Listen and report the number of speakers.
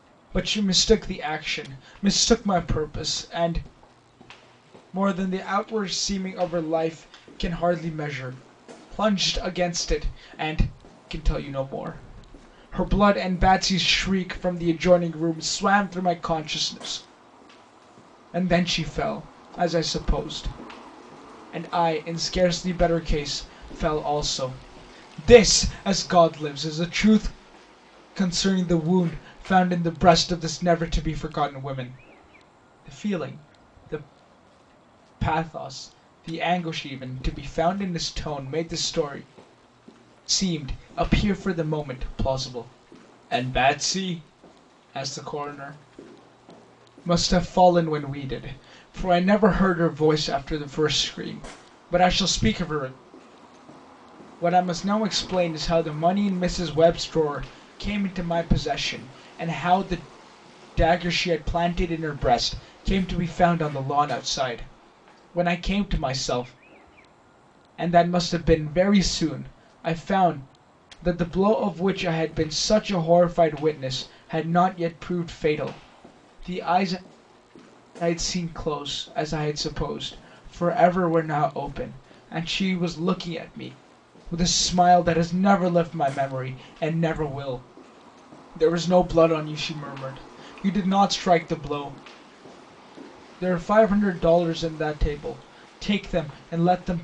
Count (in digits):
1